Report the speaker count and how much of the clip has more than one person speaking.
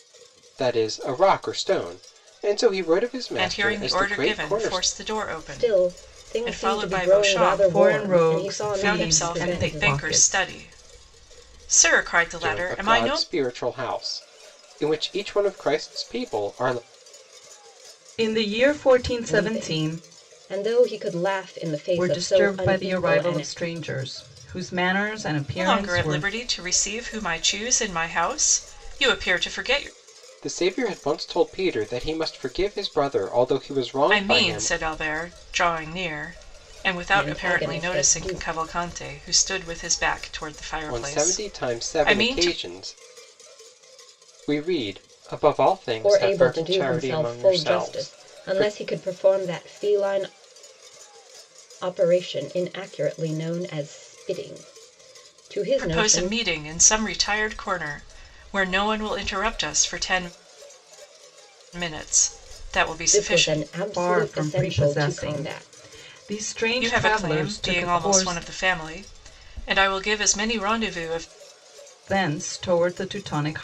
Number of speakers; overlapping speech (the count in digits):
4, about 30%